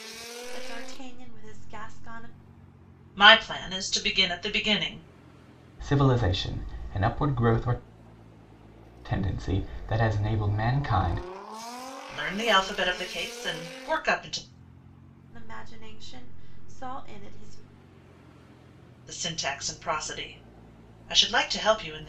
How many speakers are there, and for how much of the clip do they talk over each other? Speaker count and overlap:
3, no overlap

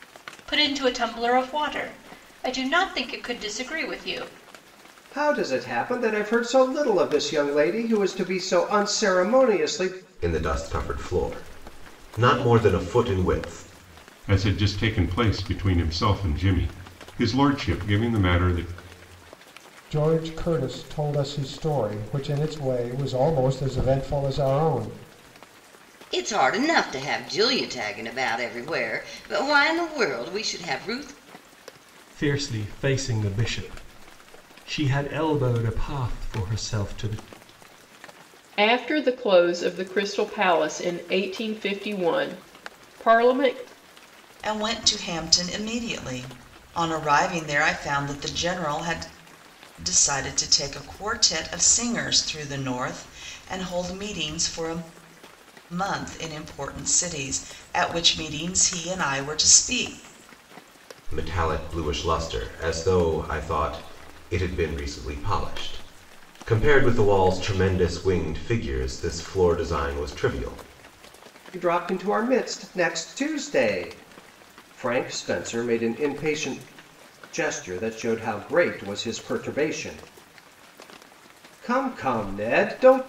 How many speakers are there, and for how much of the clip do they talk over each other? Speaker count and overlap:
9, no overlap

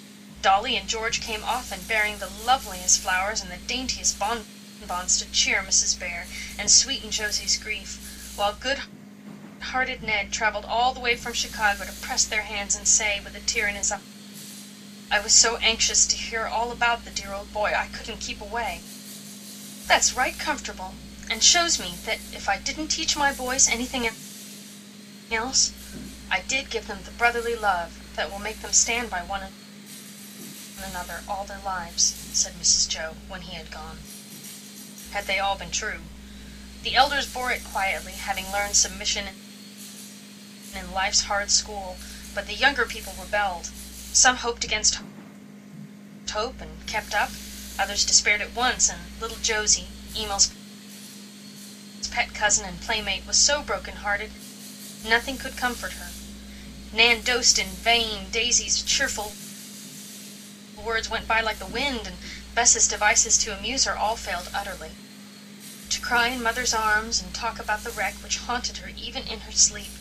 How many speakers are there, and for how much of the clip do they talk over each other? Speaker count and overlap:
1, no overlap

